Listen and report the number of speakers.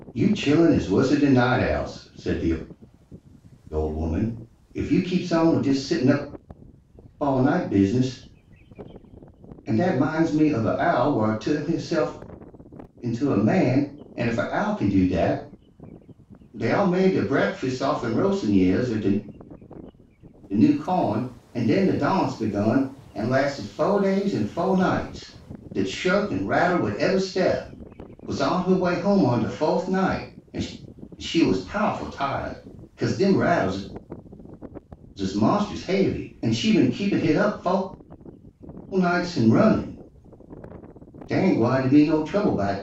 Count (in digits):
1